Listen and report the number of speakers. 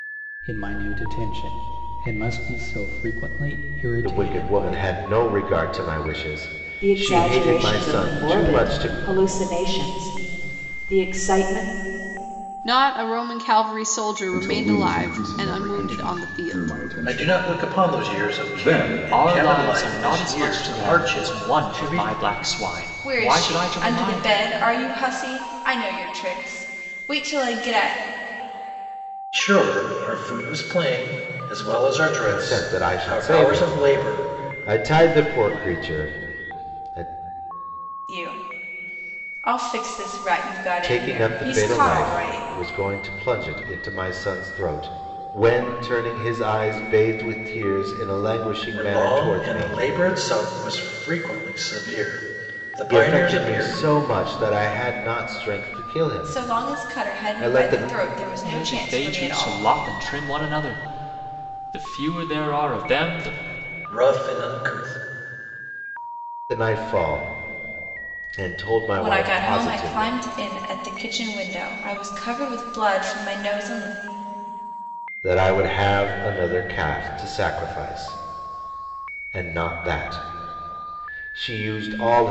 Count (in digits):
8